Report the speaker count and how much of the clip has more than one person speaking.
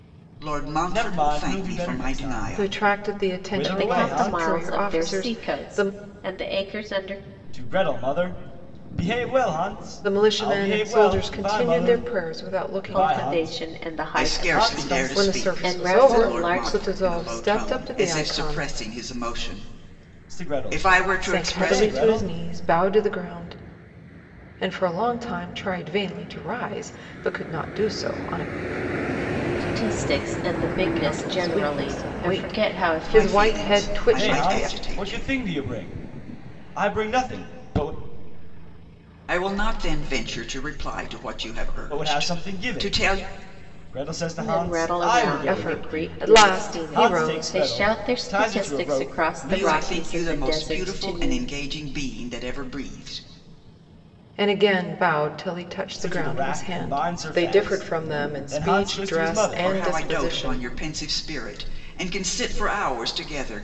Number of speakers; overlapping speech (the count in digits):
4, about 52%